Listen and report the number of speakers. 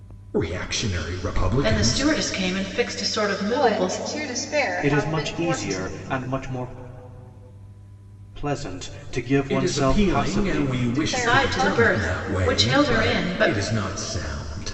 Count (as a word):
four